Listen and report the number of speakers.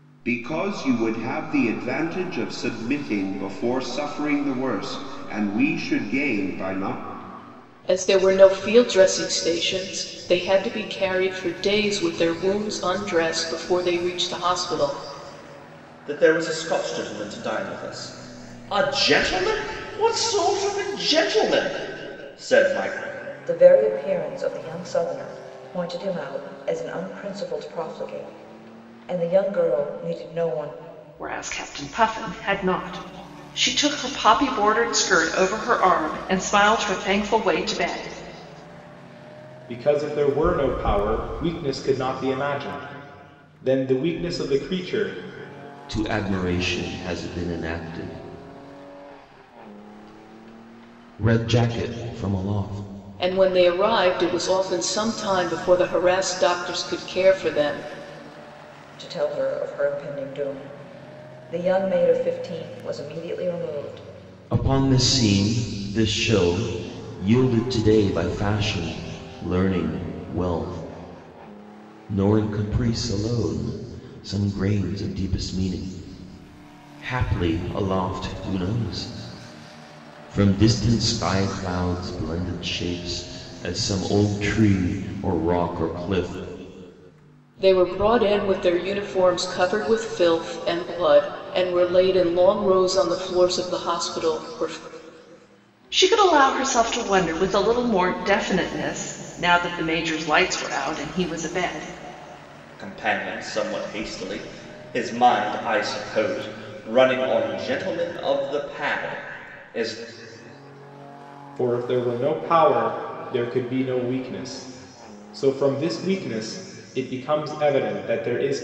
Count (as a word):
seven